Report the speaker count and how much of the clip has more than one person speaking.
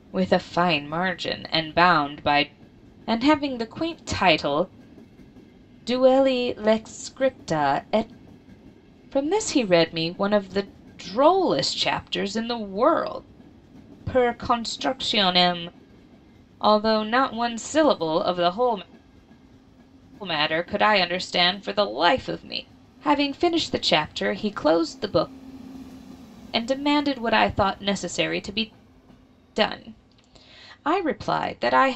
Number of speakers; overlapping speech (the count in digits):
1, no overlap